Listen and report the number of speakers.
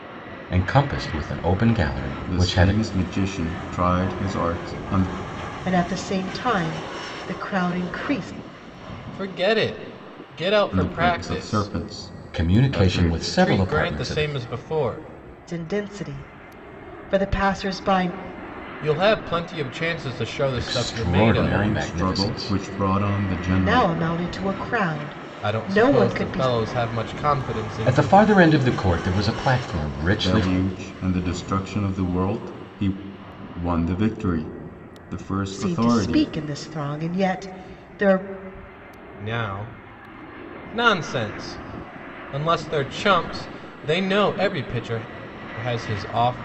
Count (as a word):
four